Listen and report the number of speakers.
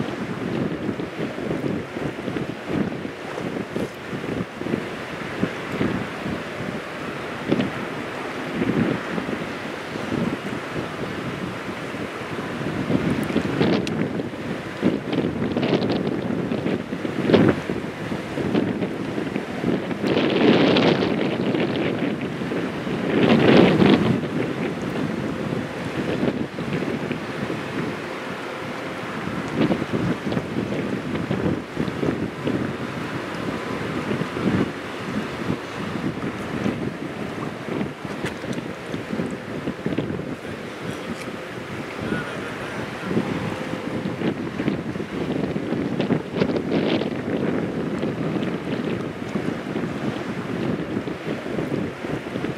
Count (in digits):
0